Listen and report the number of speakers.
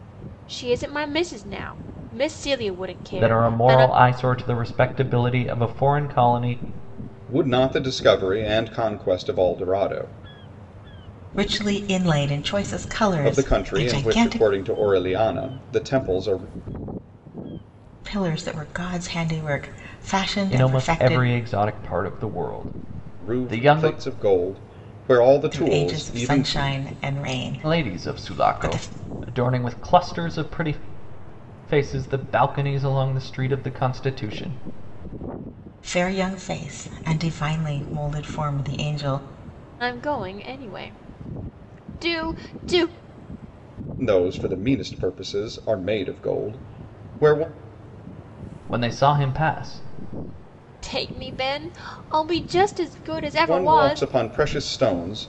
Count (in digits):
4